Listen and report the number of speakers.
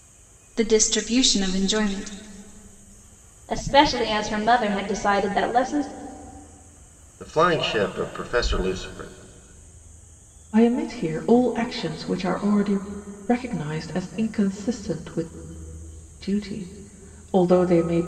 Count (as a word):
four